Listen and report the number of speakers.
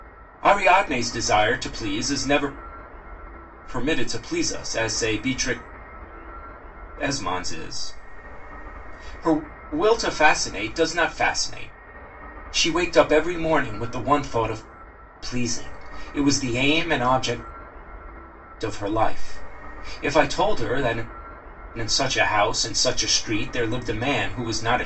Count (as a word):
one